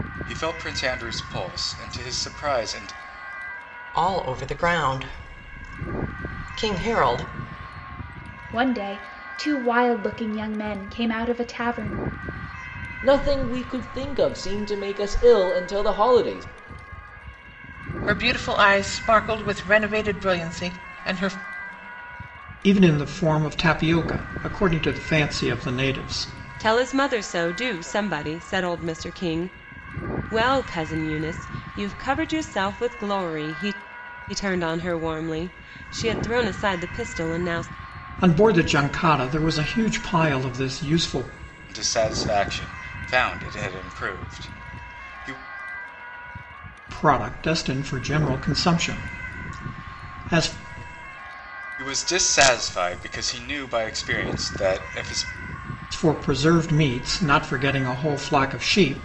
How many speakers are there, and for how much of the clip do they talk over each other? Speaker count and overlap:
seven, no overlap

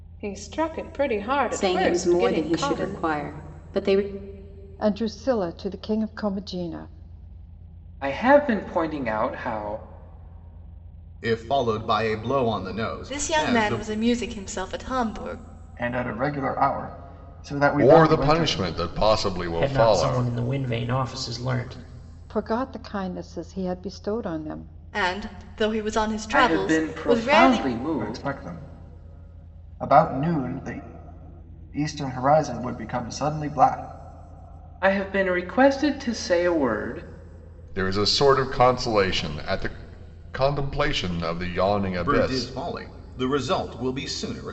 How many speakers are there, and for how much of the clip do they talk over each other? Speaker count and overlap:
nine, about 13%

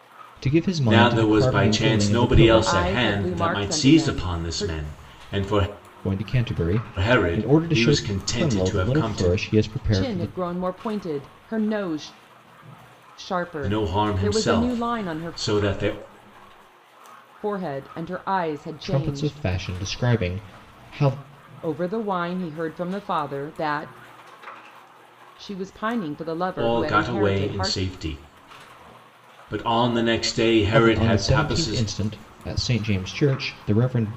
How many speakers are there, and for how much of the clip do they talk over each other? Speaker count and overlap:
three, about 34%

